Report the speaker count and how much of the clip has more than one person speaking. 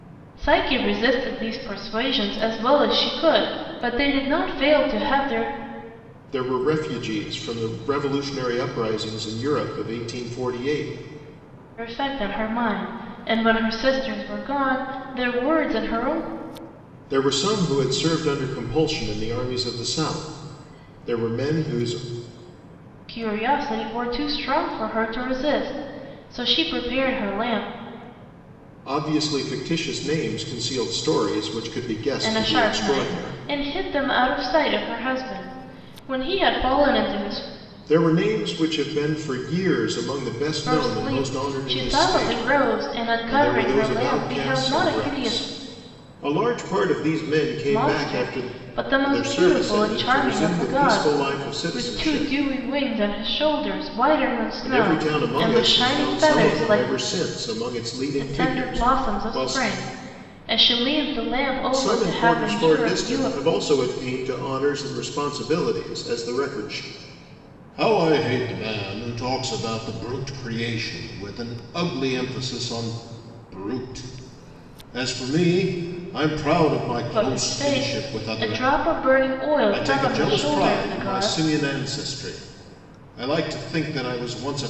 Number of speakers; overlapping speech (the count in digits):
2, about 21%